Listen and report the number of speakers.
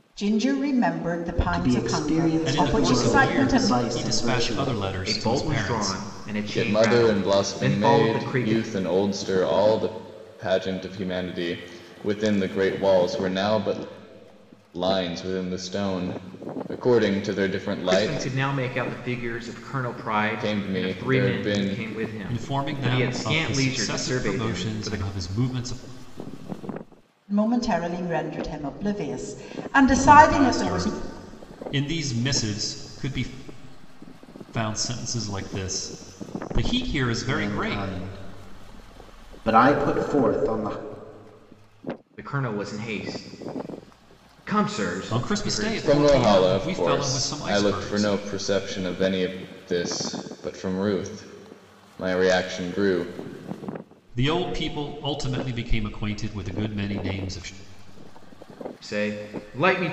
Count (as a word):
five